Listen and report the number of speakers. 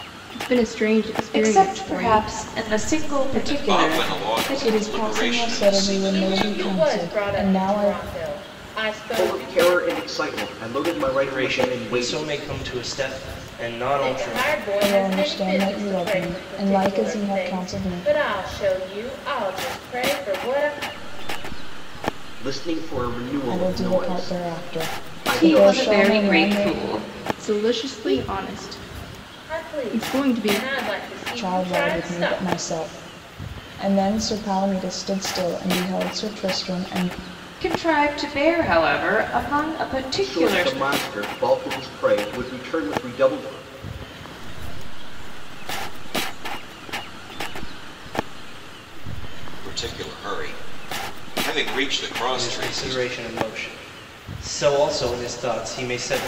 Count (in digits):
8